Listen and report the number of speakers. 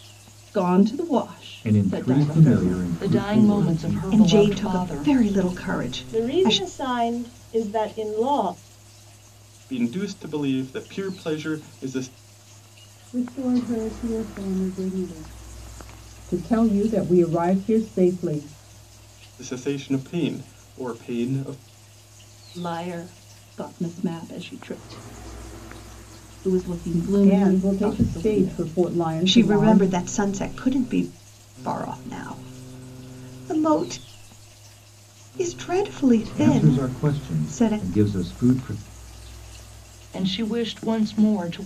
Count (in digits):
8